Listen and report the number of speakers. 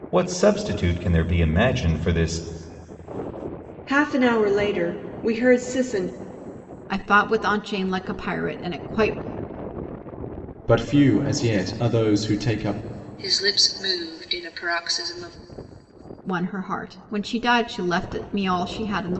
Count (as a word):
five